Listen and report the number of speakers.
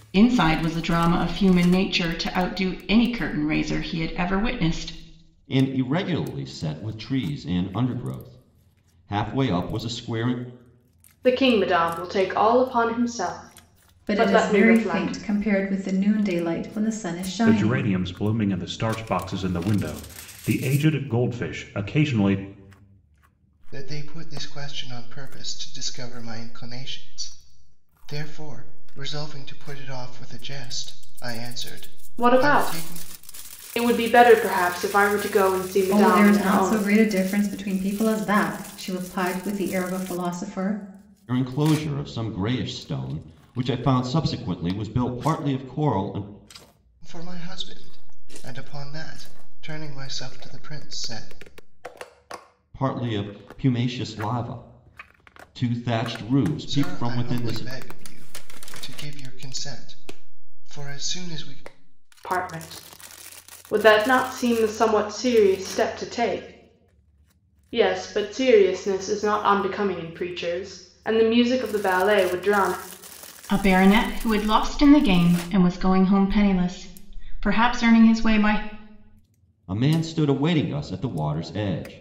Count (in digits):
6